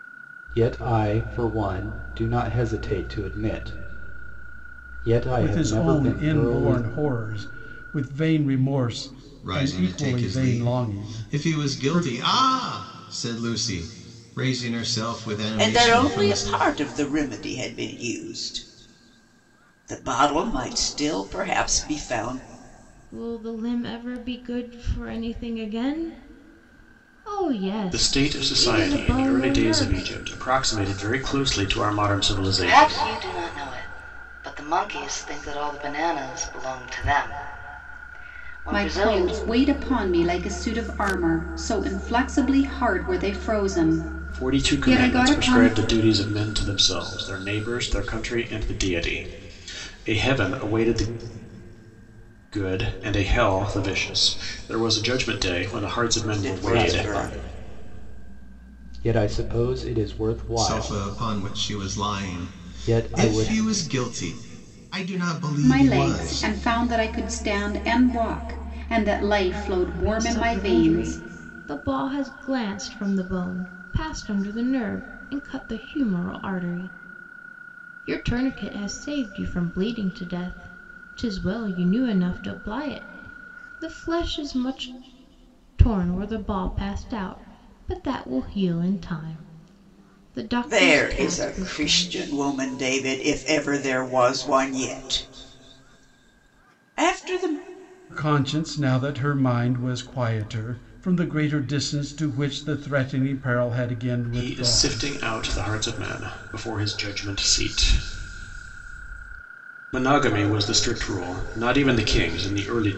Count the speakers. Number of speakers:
eight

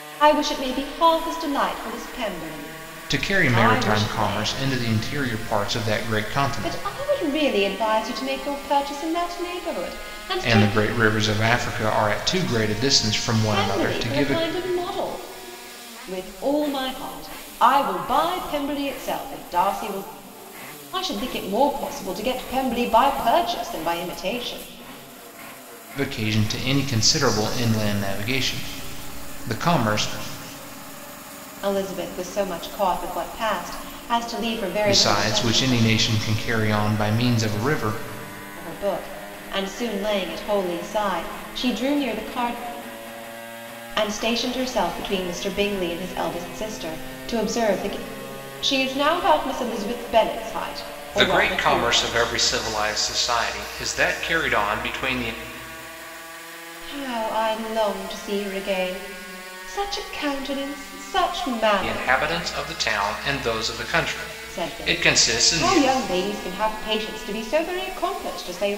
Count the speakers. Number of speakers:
two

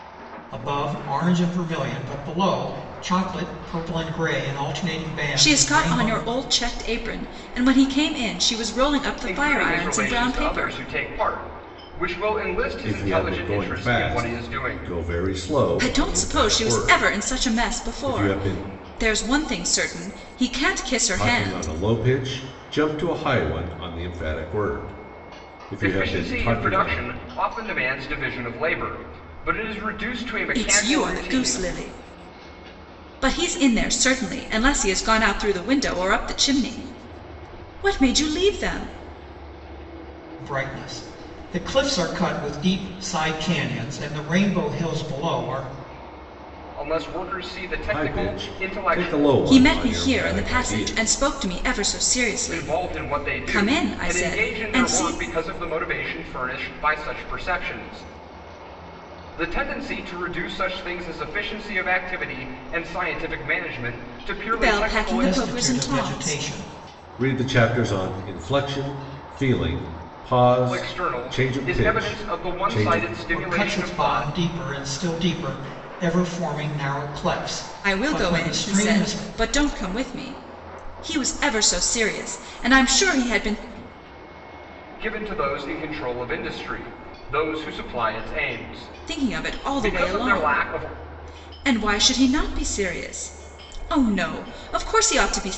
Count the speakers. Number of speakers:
four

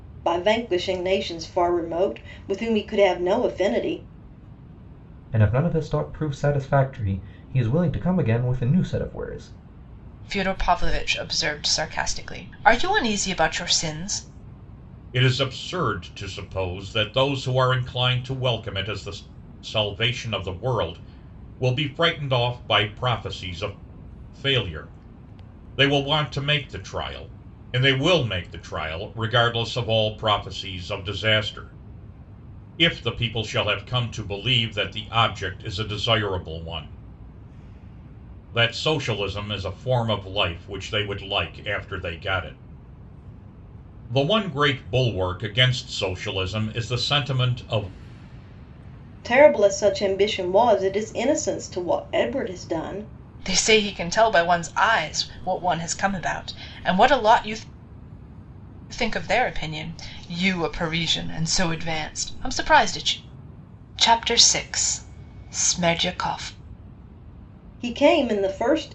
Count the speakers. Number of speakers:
four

